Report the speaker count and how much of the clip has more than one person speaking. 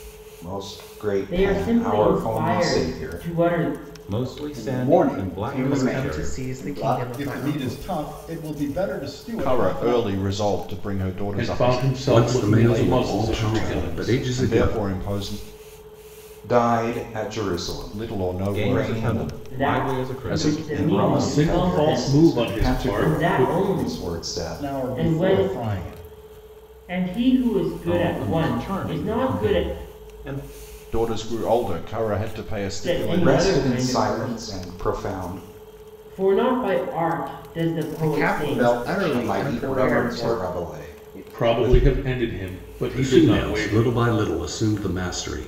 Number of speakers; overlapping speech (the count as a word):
nine, about 55%